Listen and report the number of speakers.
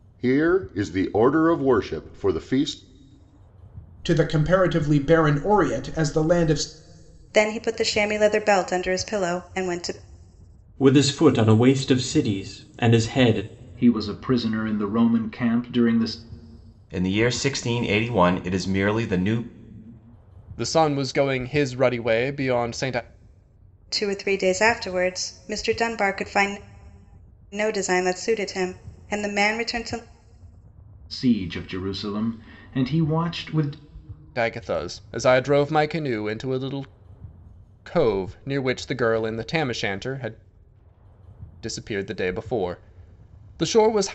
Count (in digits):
7